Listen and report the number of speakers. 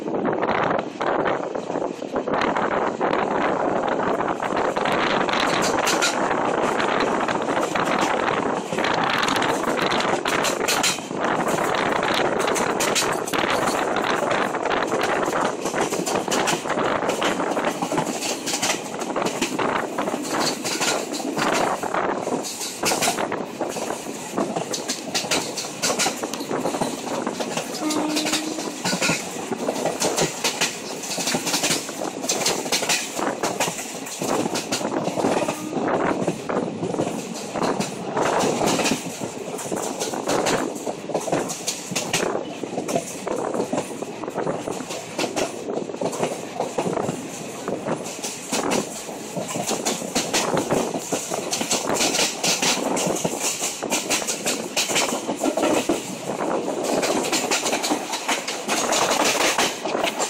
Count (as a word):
zero